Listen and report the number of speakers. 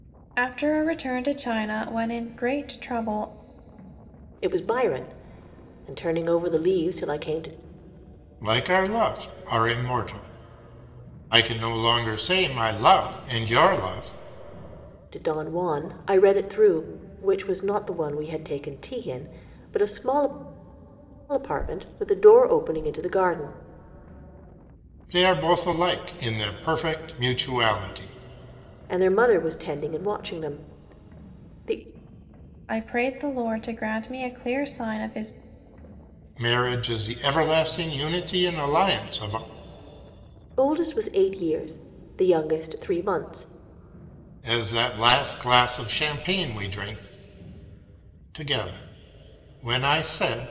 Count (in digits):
3